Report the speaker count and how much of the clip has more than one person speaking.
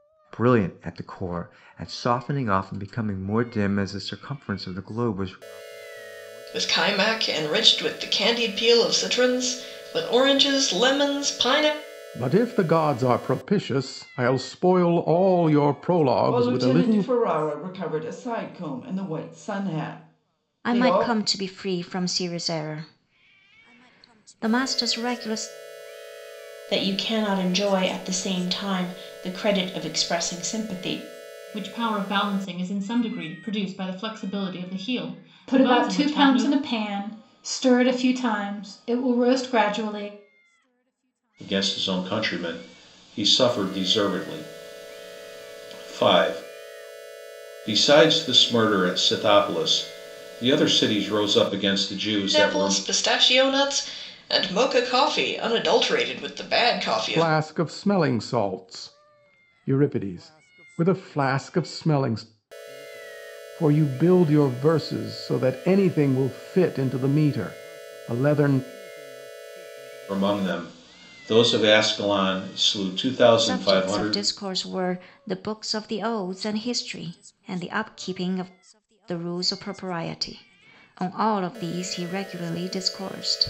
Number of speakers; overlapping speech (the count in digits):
9, about 5%